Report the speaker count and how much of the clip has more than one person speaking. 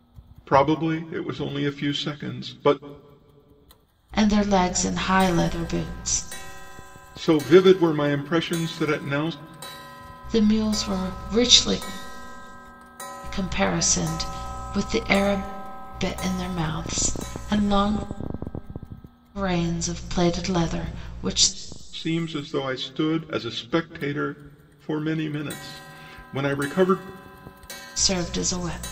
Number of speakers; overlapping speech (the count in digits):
2, no overlap